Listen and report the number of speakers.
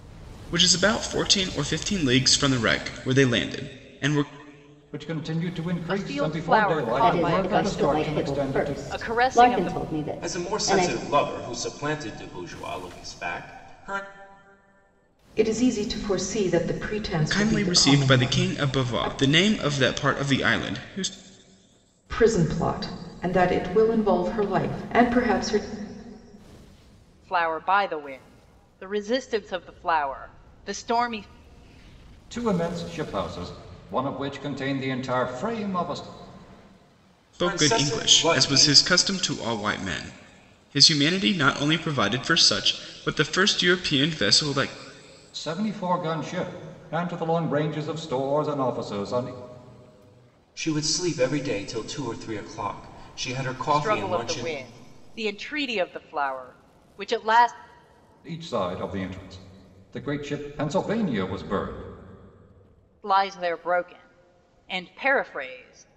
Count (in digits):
6